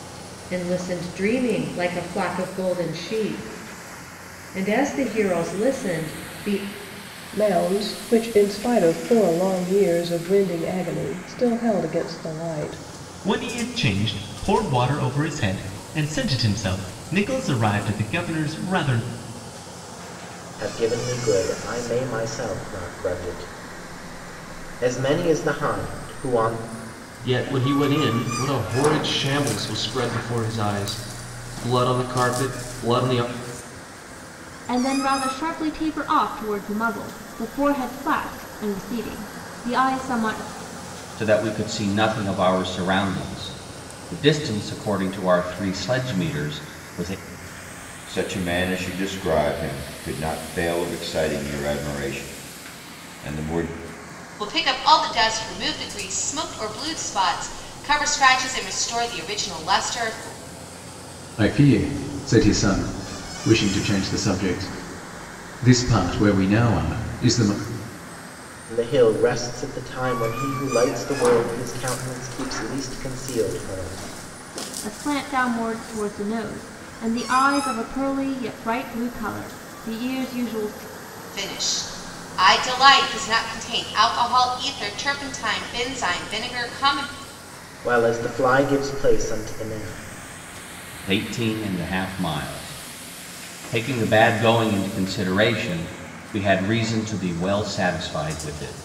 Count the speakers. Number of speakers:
ten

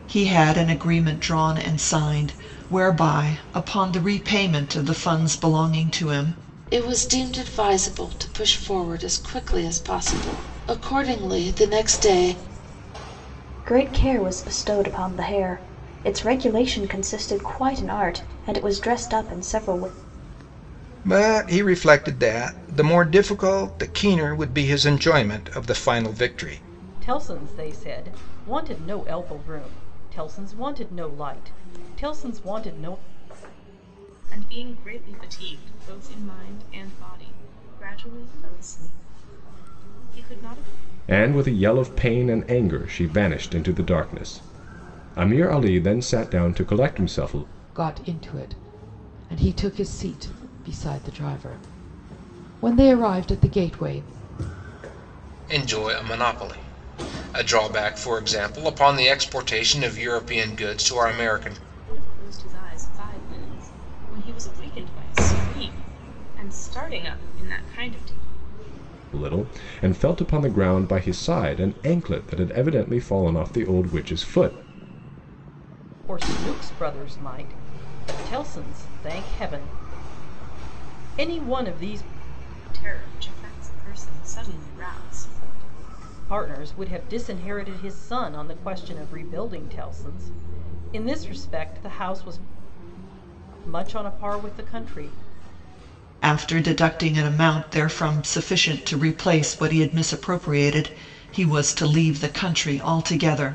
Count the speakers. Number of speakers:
nine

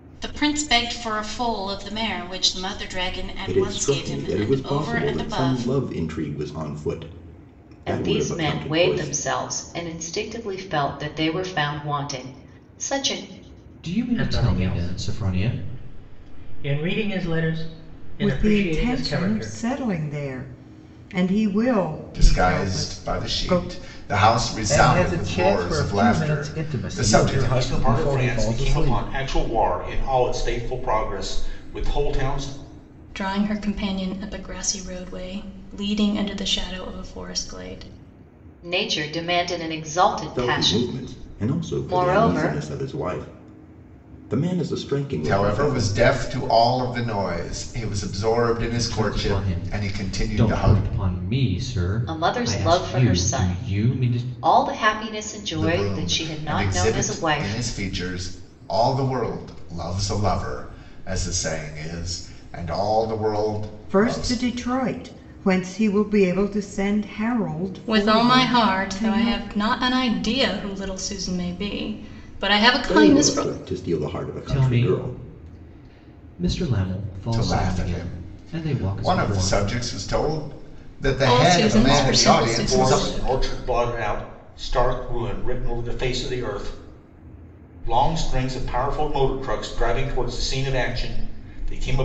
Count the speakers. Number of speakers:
ten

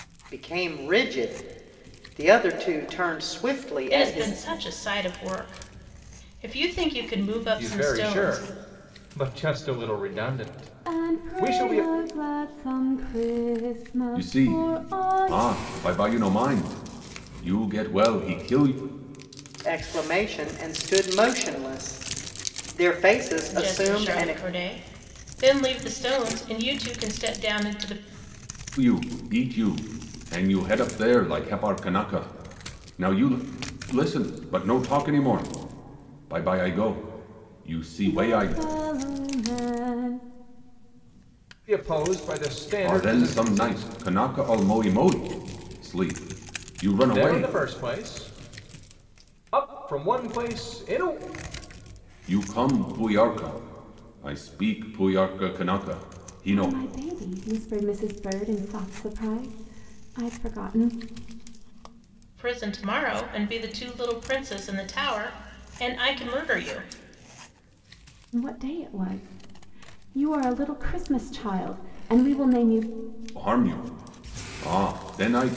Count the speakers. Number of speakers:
five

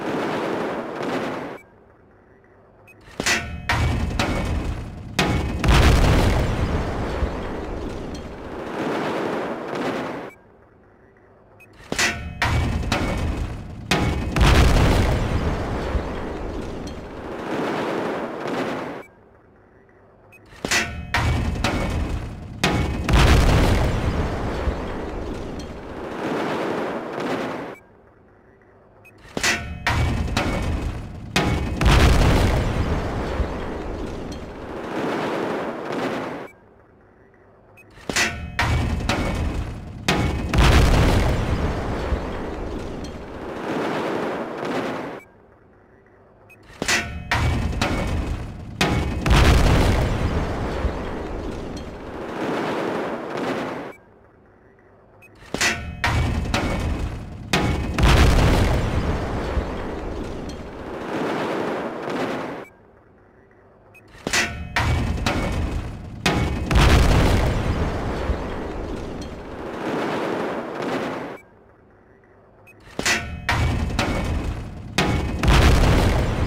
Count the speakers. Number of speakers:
zero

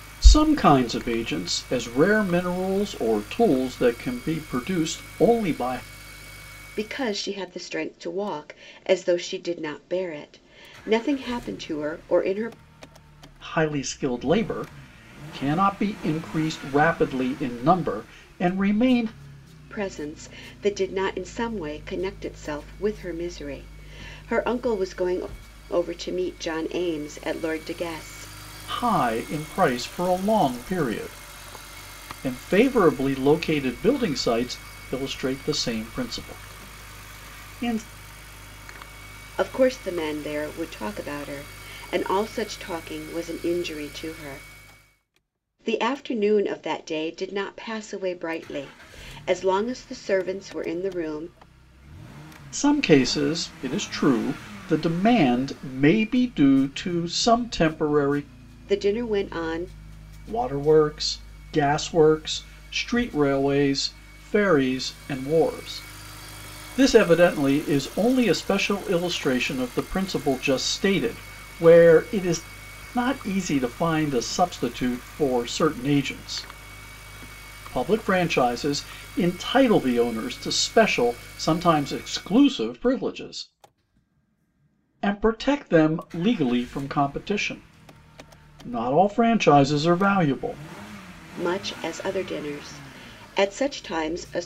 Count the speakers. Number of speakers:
two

